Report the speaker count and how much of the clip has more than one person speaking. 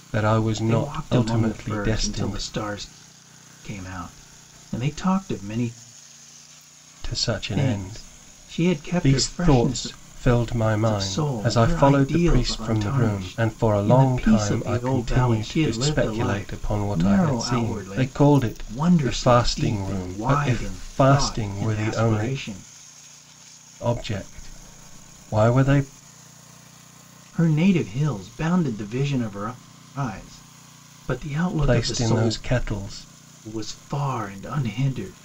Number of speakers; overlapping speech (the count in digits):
2, about 44%